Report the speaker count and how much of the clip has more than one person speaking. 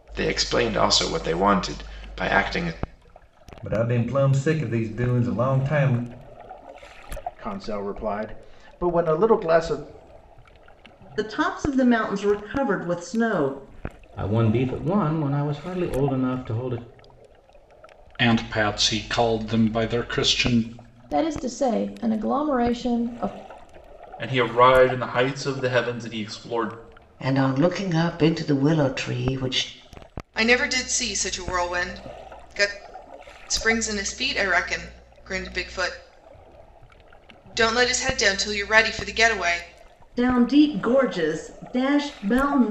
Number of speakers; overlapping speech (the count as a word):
ten, no overlap